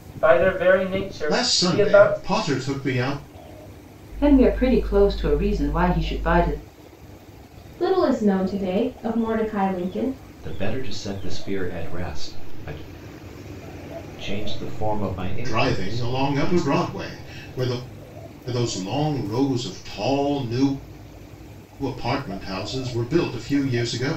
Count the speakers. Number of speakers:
five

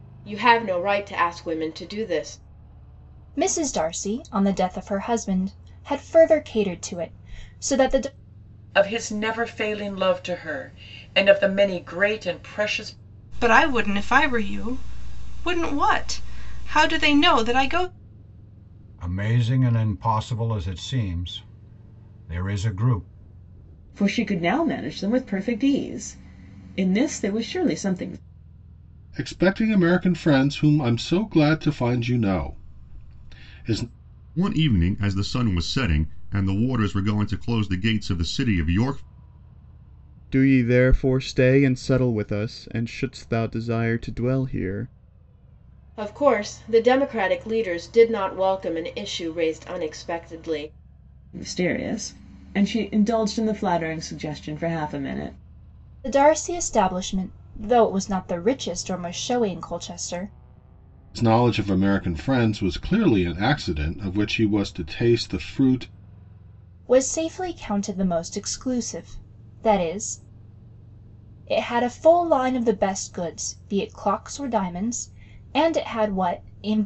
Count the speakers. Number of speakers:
nine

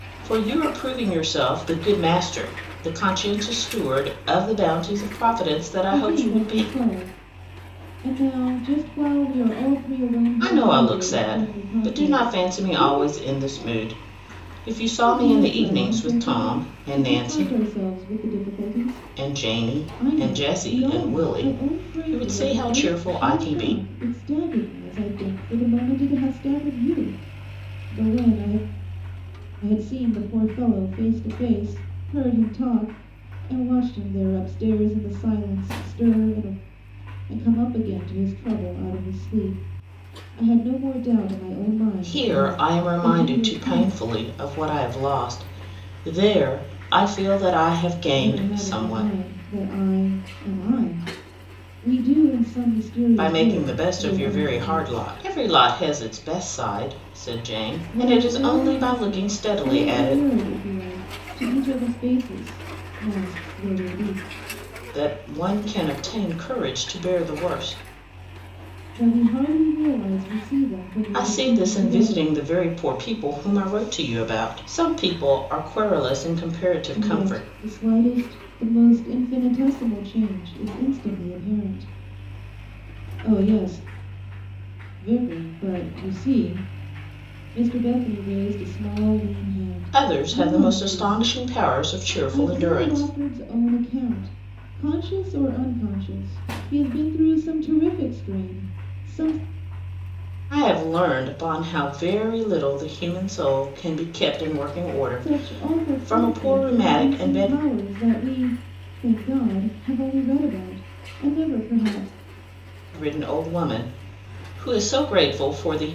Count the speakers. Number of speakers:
two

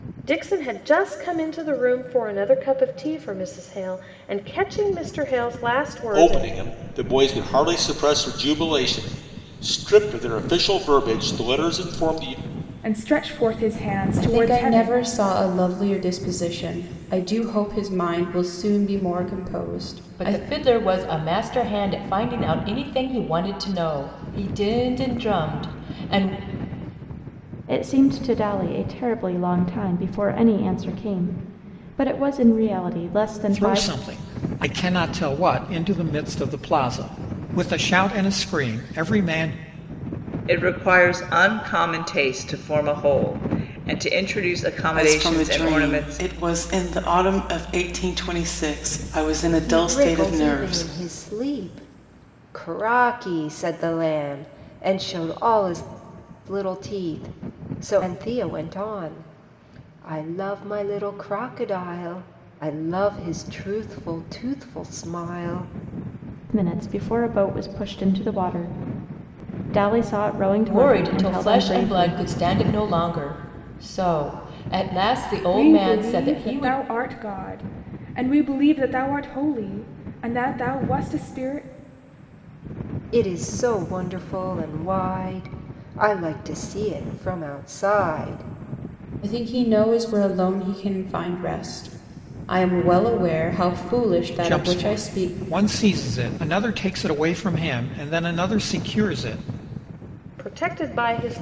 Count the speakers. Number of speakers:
ten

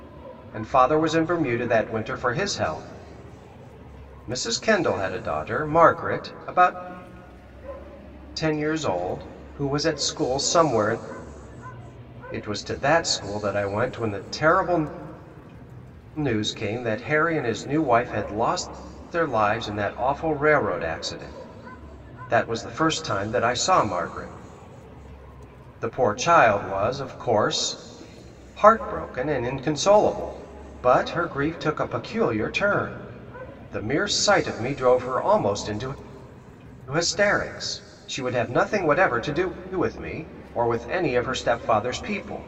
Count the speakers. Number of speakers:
one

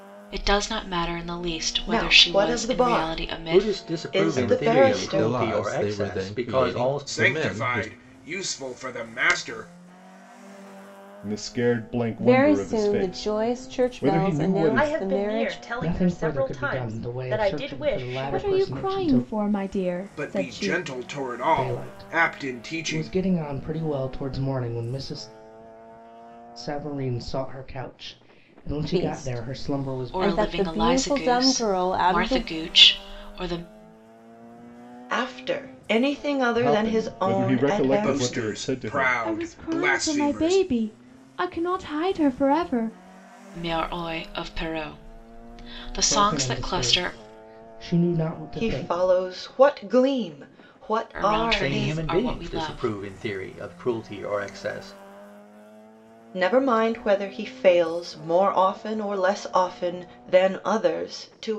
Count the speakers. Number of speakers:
ten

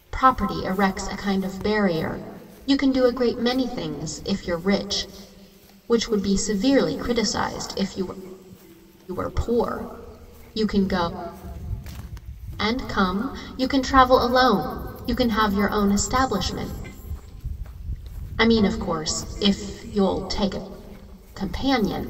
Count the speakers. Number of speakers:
one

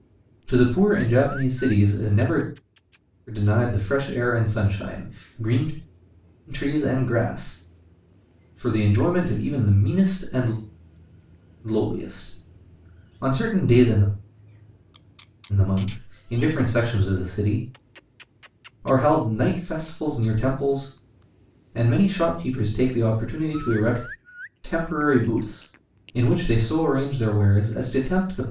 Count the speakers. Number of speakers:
one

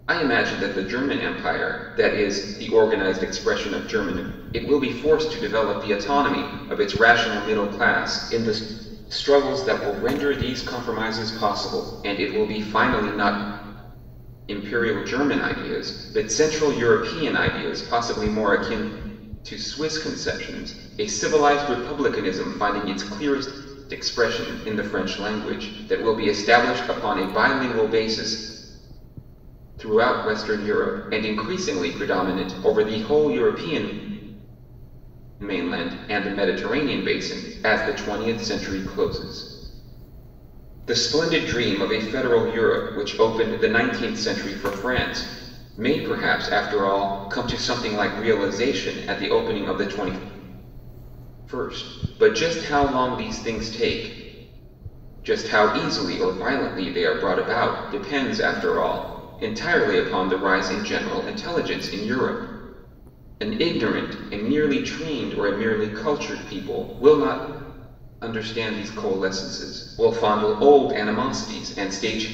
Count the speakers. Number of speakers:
one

